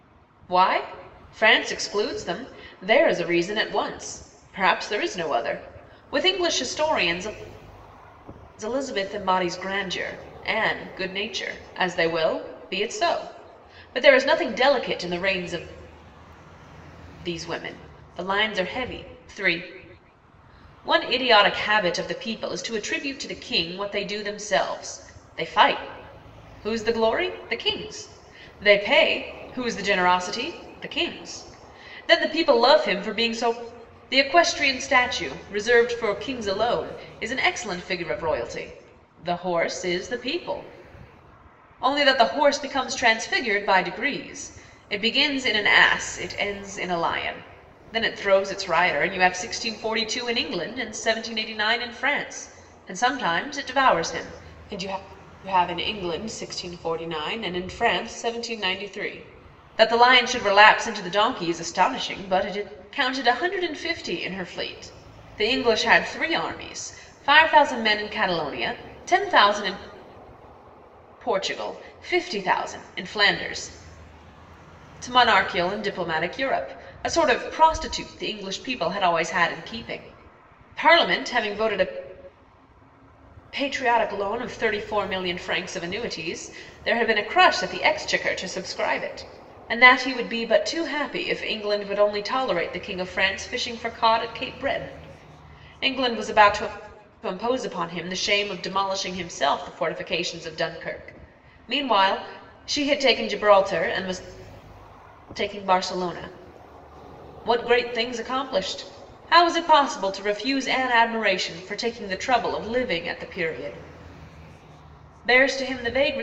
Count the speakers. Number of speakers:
one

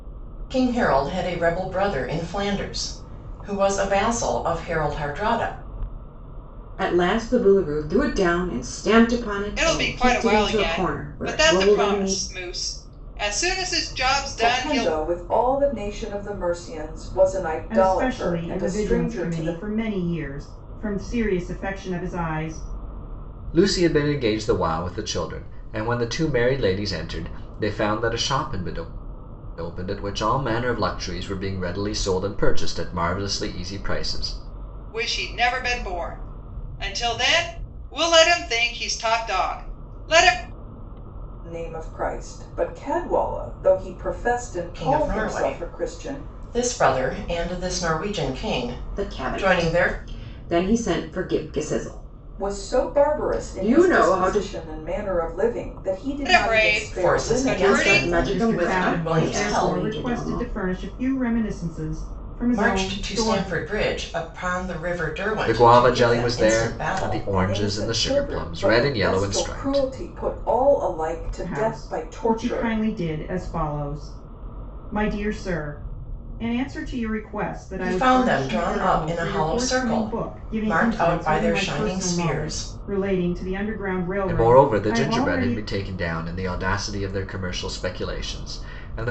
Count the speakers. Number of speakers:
six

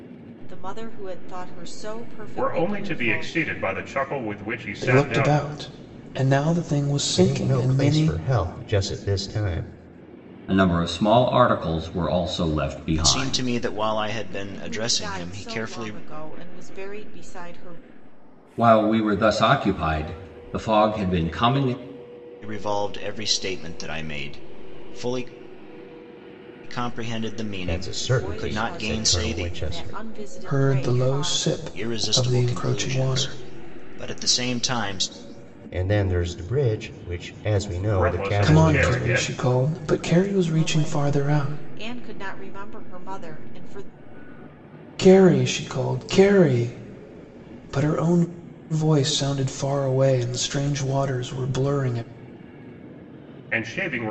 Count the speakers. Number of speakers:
six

